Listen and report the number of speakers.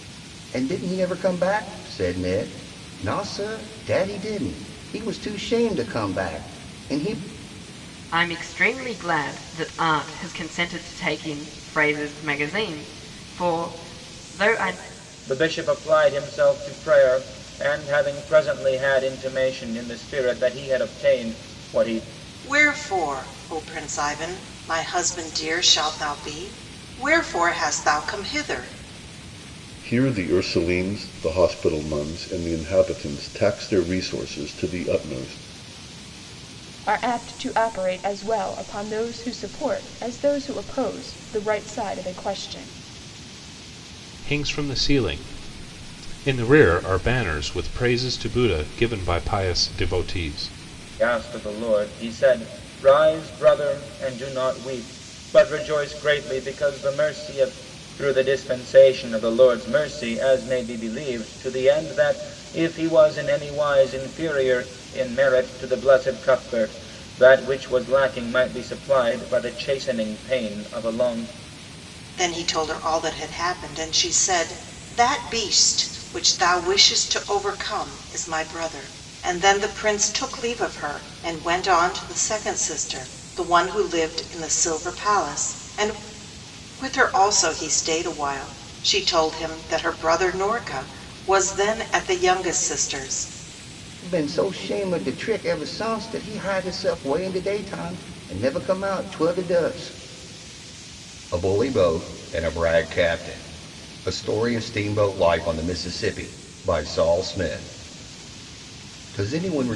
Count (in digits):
7